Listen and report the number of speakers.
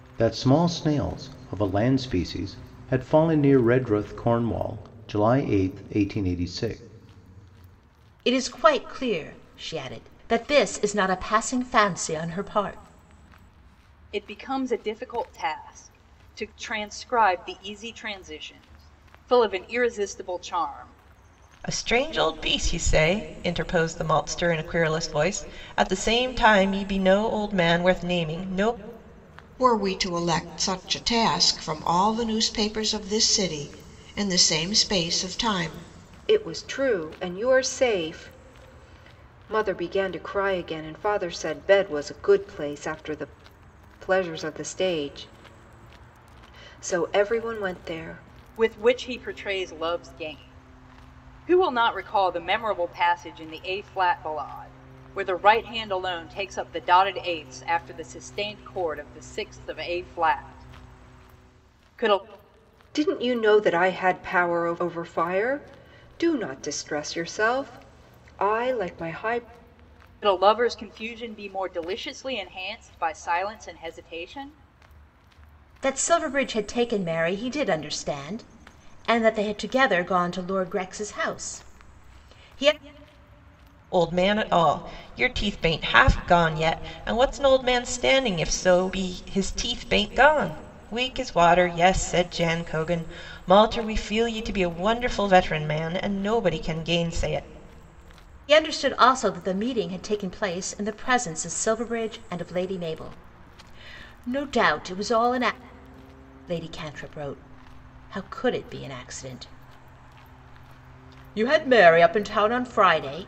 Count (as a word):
six